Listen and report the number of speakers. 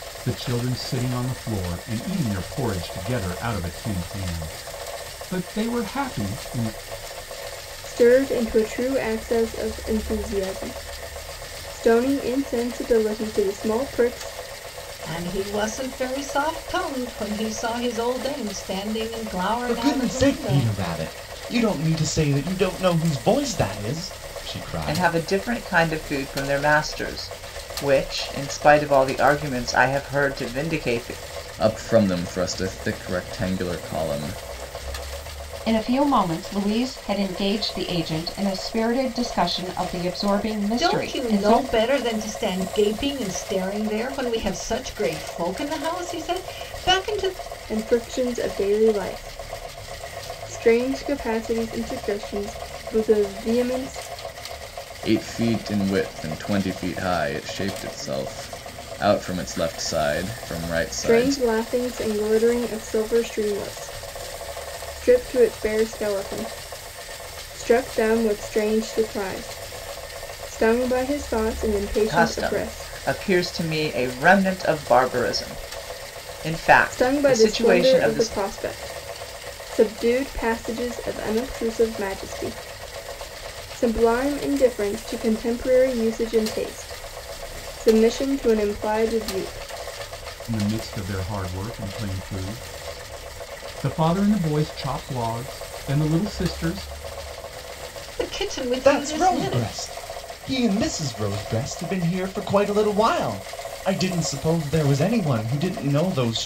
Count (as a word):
seven